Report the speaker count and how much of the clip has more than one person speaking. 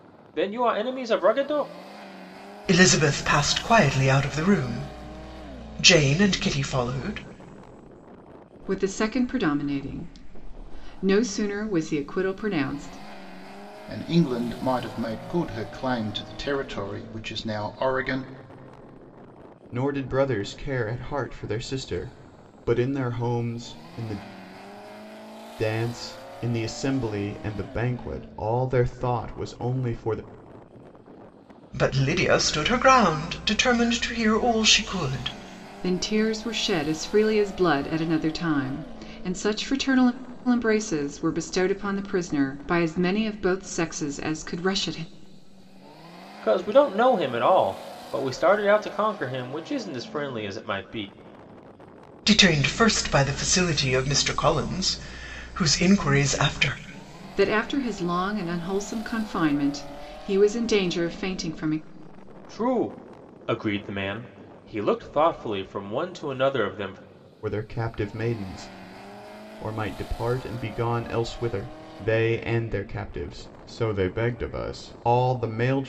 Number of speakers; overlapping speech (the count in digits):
5, no overlap